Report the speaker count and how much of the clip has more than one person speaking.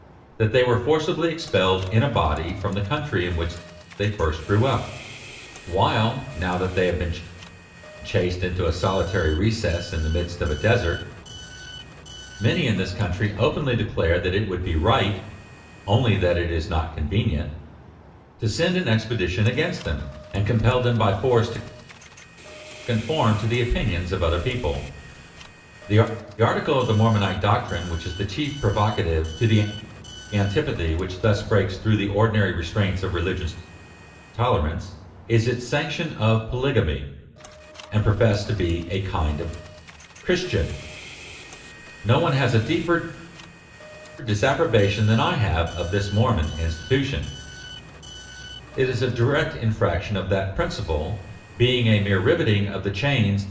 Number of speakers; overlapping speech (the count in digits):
1, no overlap